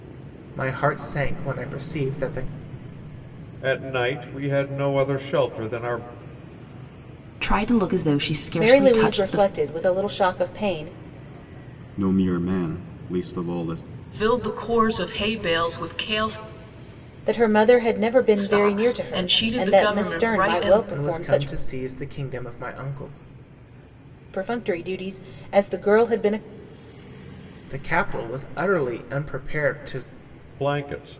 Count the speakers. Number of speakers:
6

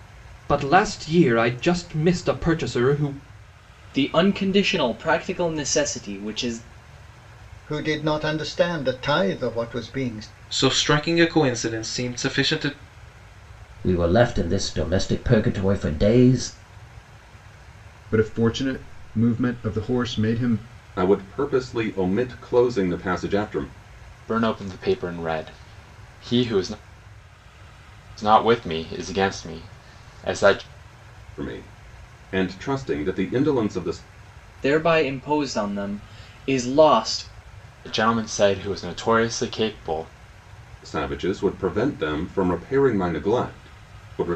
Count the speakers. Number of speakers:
8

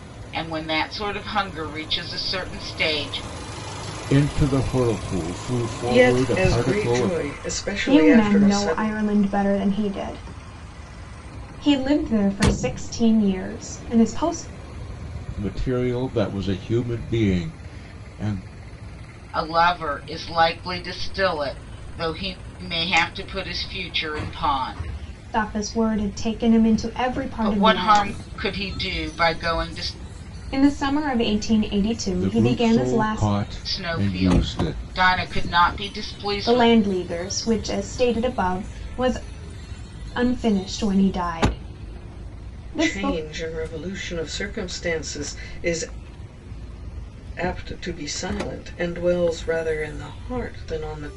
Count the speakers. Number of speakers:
4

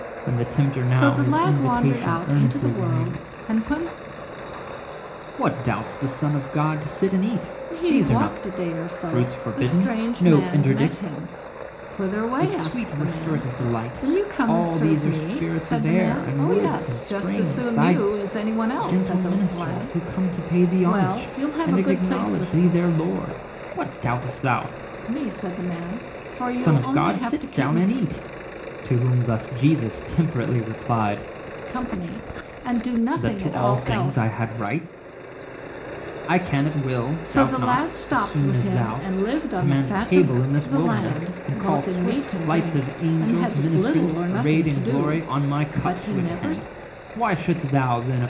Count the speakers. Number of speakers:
2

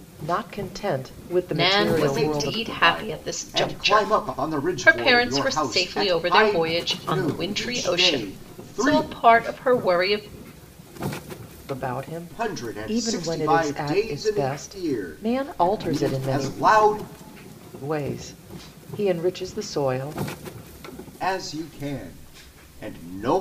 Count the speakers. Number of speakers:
3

